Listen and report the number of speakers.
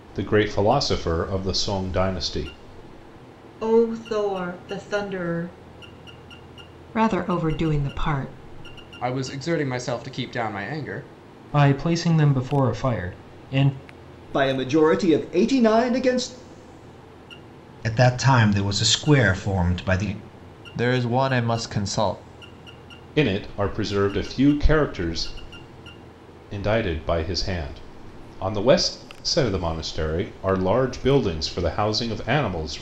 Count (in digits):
8